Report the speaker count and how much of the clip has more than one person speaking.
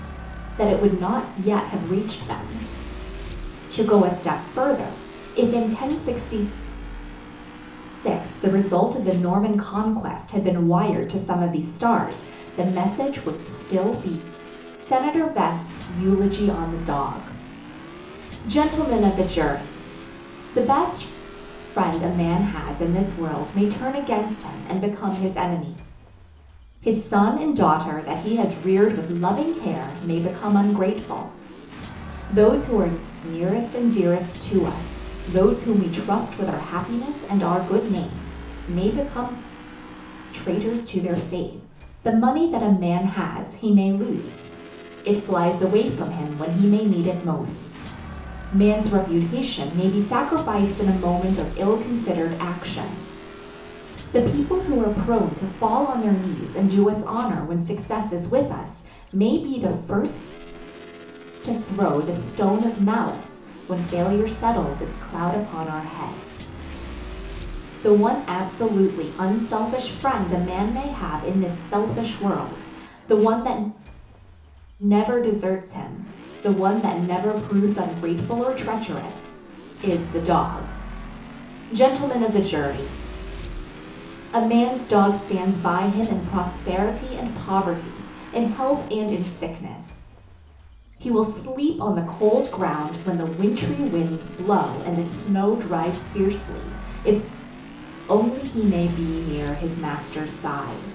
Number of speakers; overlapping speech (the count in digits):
1, no overlap